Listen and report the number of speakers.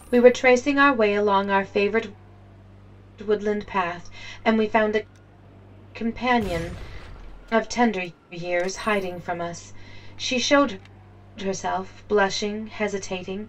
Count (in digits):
1